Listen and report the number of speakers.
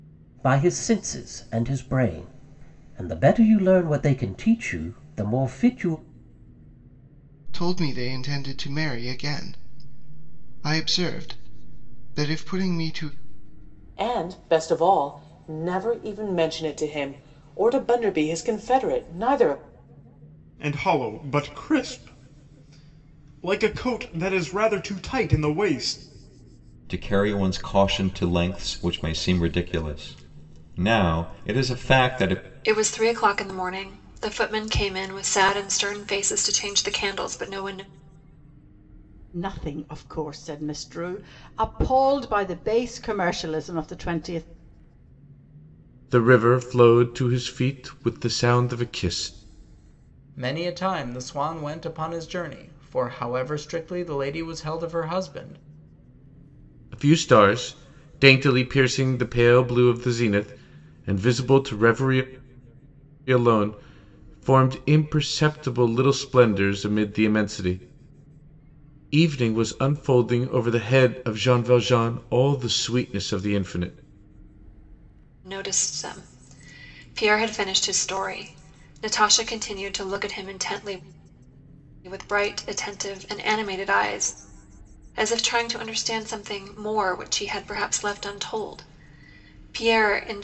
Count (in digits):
9